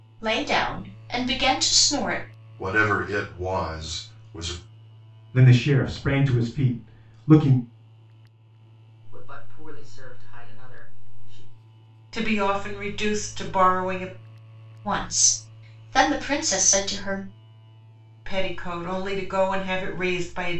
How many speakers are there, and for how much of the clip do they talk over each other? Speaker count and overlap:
5, no overlap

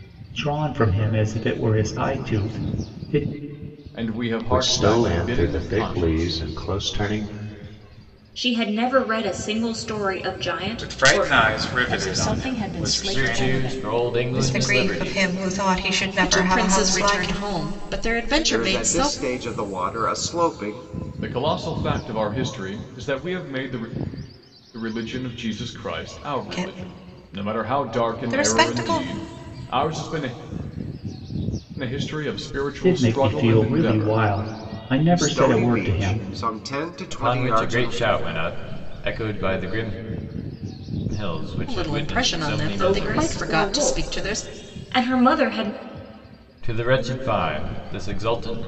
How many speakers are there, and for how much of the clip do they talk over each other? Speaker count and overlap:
10, about 34%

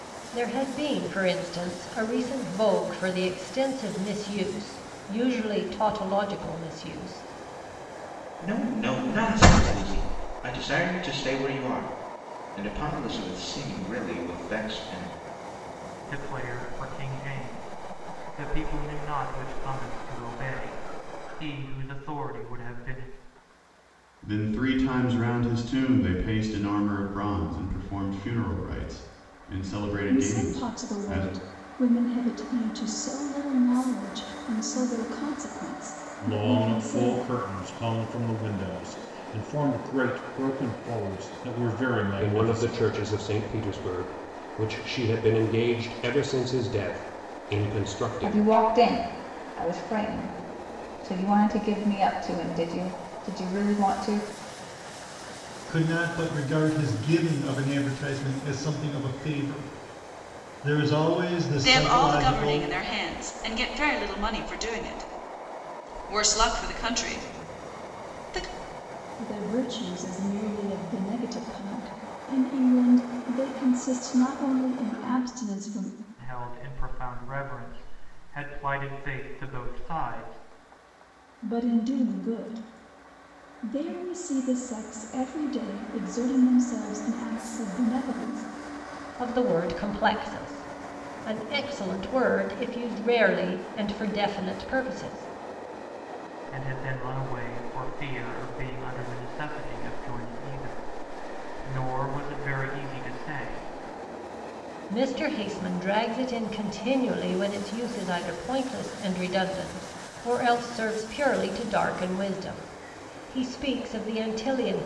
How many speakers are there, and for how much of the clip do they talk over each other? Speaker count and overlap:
10, about 4%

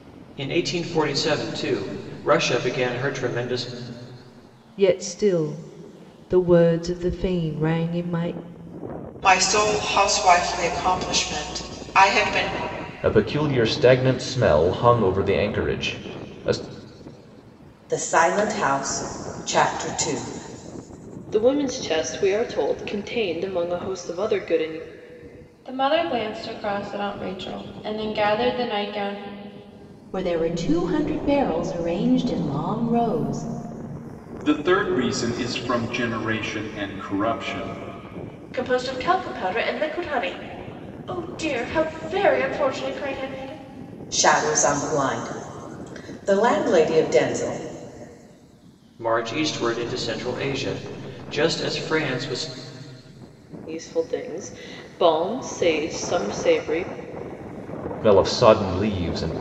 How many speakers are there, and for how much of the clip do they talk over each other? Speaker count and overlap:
10, no overlap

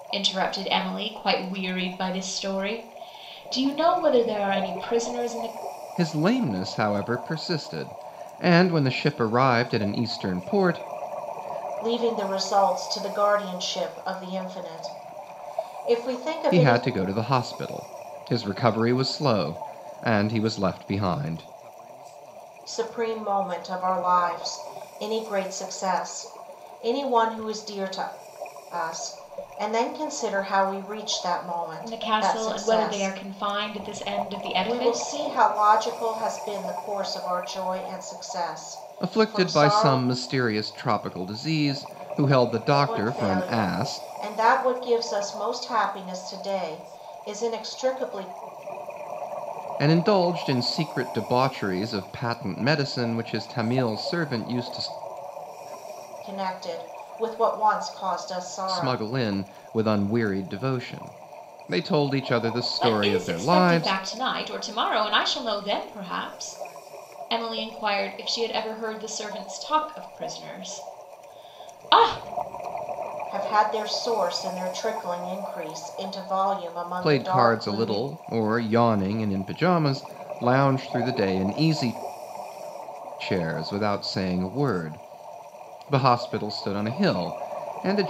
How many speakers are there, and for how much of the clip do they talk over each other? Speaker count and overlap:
3, about 8%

